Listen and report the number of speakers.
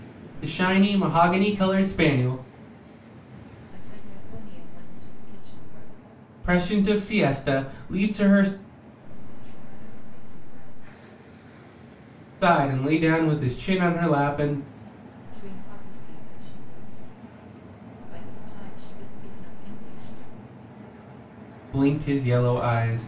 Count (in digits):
2